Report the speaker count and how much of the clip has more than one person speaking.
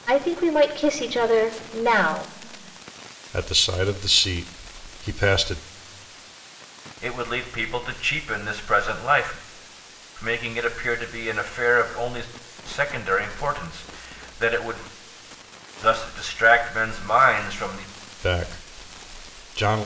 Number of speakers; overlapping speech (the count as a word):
three, no overlap